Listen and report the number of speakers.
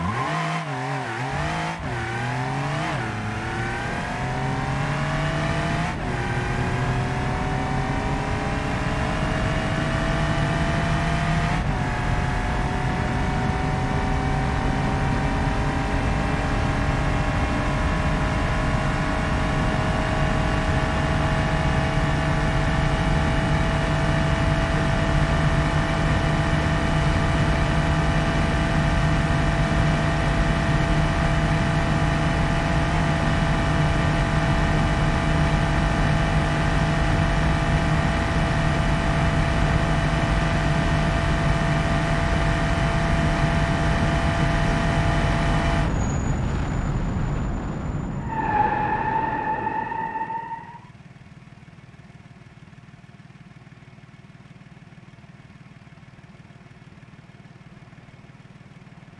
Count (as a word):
zero